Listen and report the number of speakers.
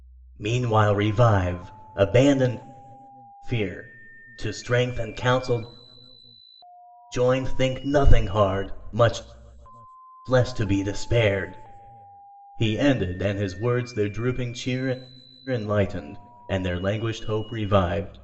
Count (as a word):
one